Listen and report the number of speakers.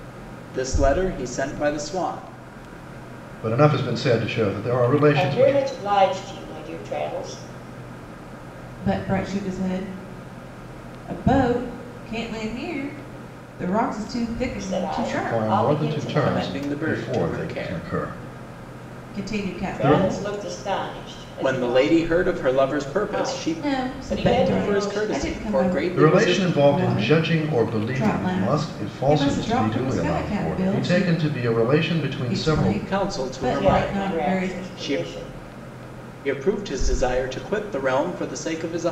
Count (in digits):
4